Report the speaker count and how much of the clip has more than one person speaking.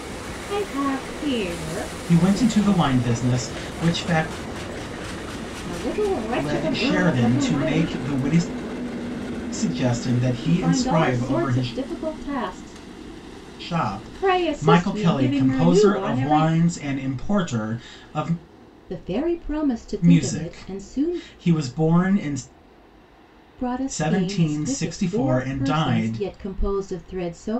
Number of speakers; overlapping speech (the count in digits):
2, about 36%